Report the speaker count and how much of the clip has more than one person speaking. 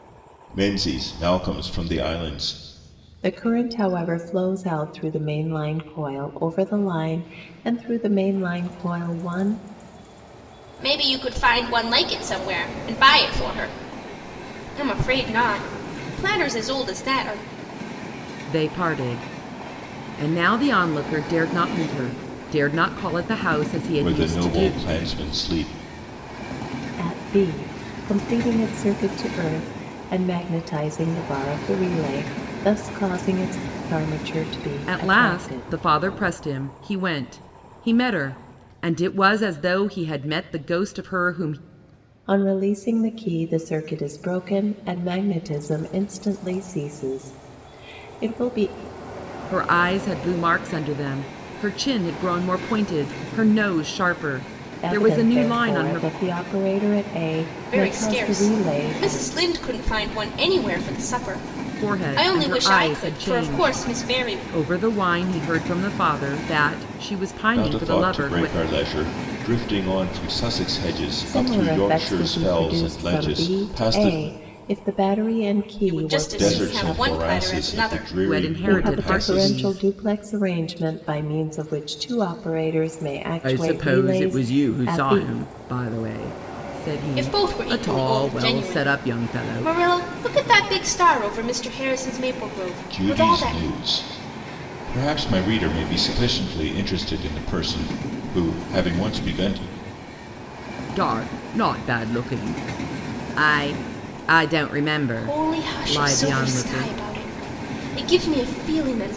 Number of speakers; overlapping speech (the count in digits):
4, about 20%